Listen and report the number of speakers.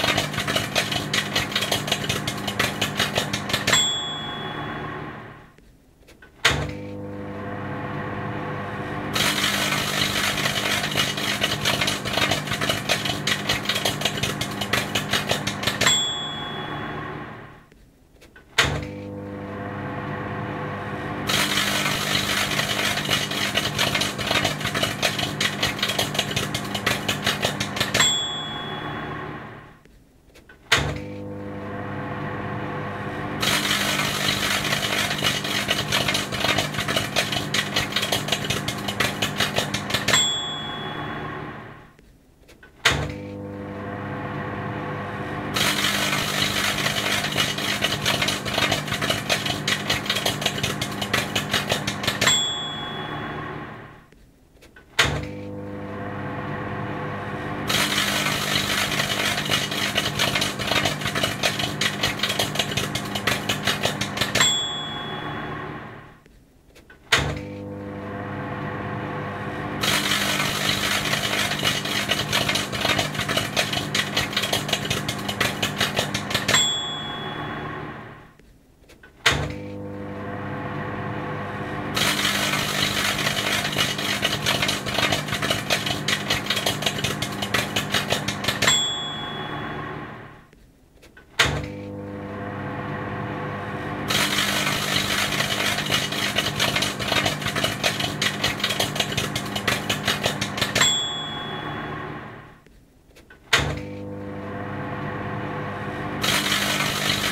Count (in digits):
0